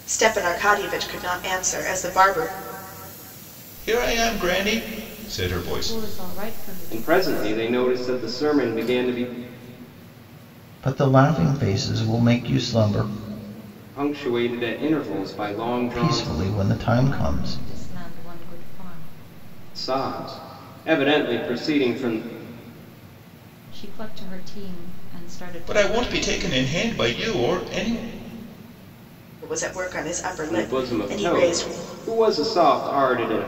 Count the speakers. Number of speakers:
five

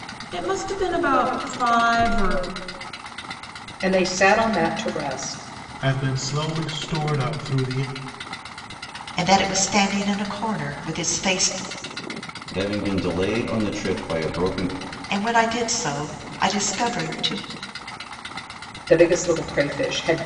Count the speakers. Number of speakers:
five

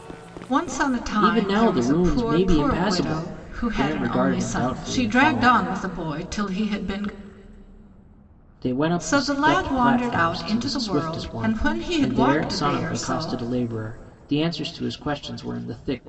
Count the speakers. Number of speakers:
two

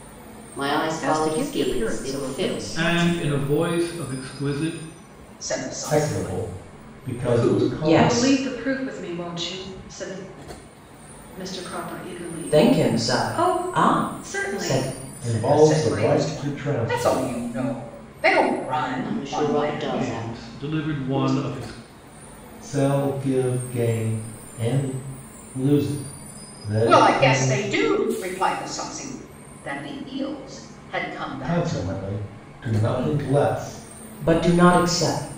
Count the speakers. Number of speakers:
seven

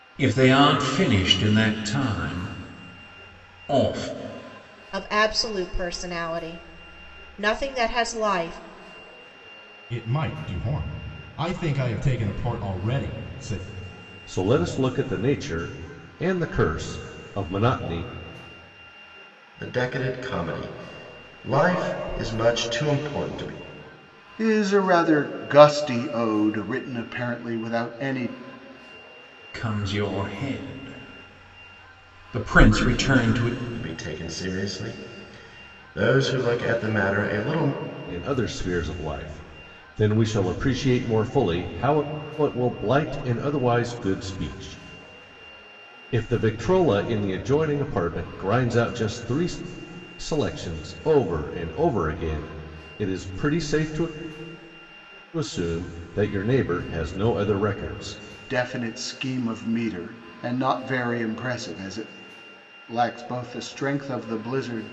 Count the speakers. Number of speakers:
six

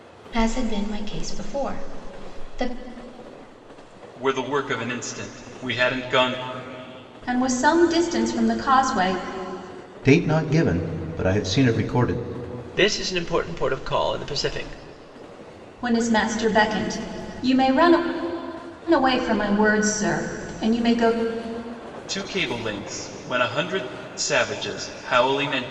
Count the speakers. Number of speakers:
five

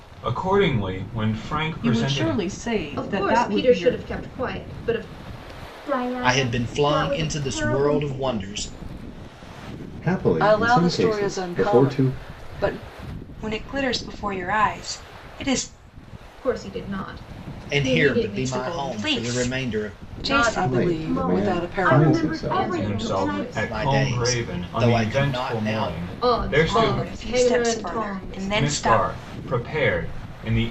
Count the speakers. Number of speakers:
eight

